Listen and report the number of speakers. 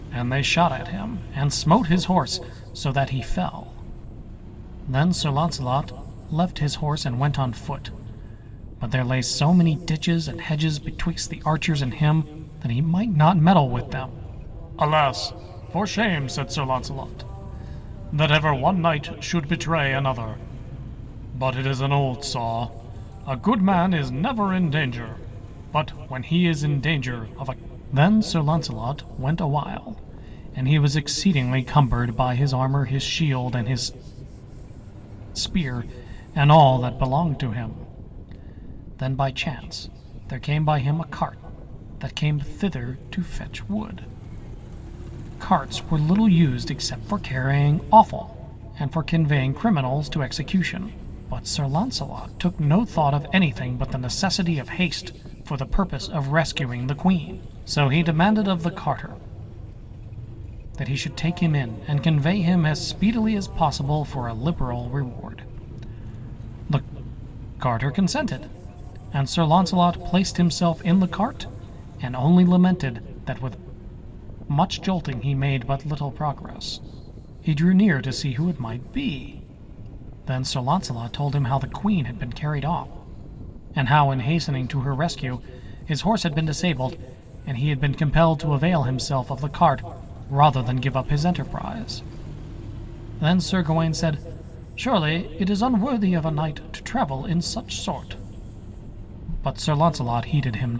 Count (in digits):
1